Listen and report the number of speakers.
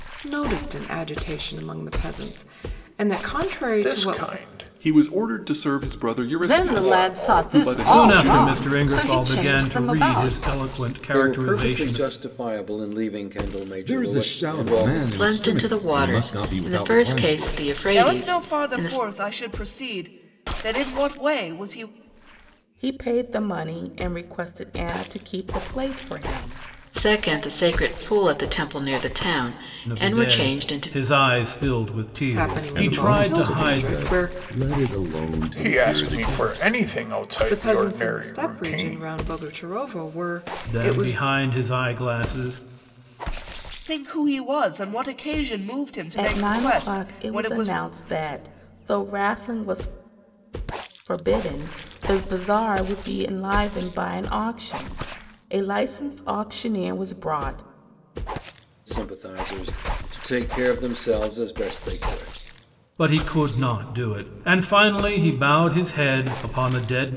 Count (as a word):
ten